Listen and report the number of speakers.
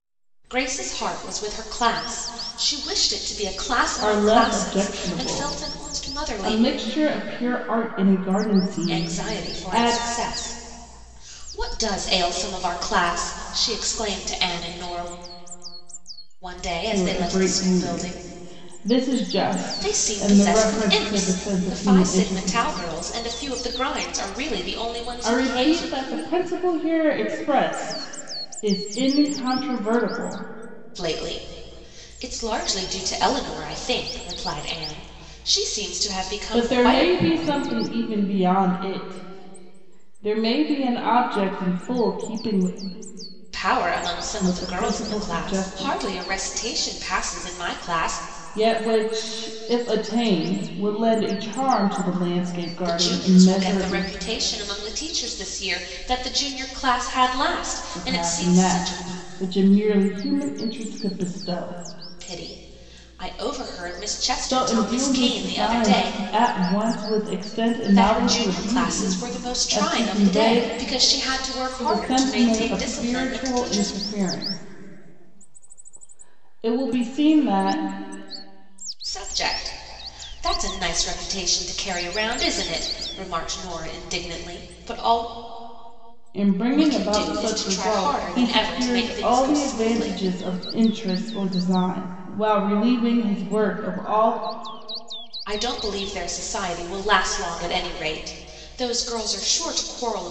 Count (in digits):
2